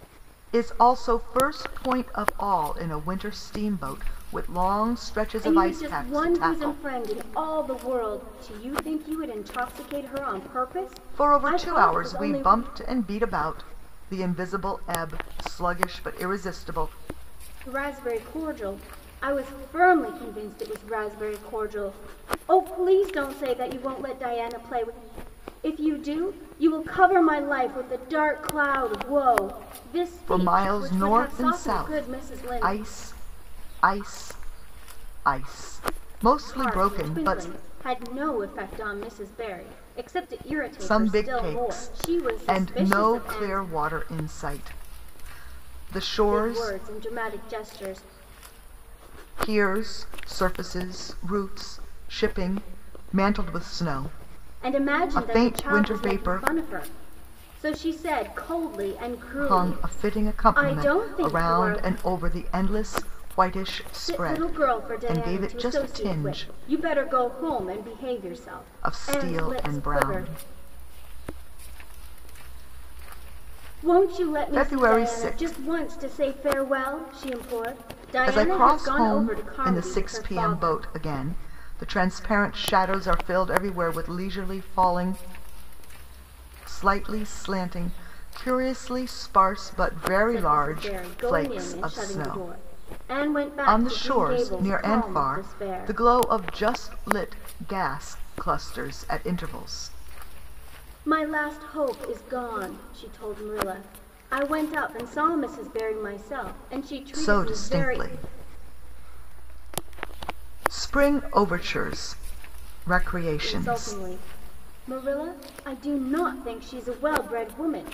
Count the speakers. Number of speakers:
two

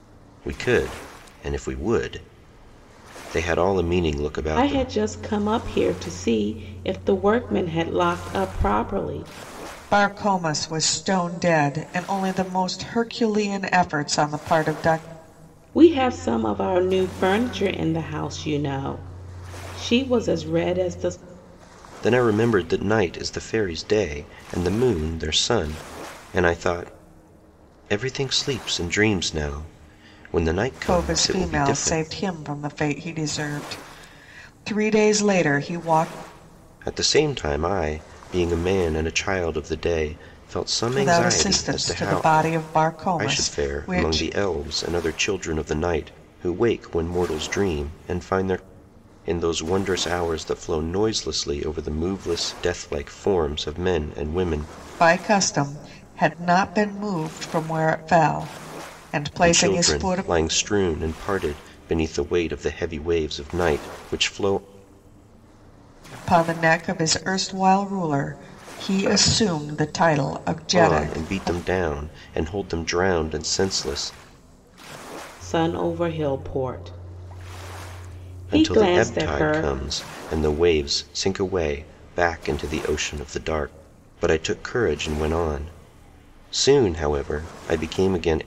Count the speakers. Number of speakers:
three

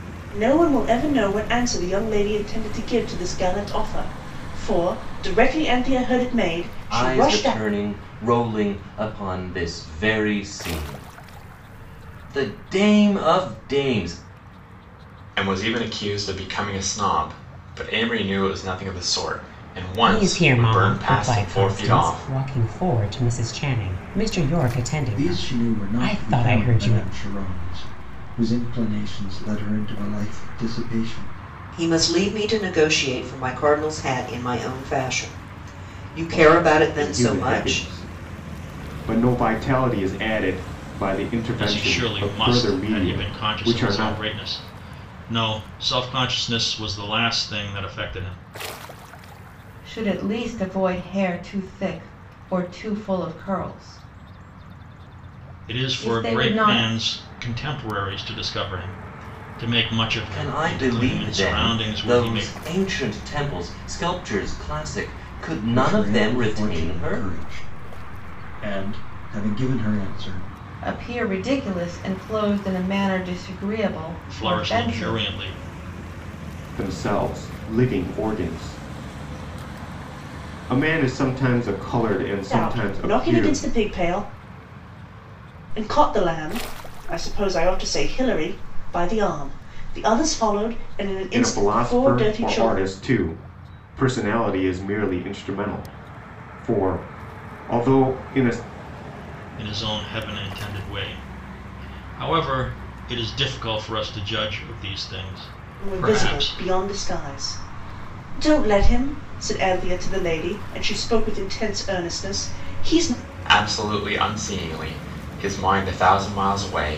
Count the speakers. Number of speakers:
nine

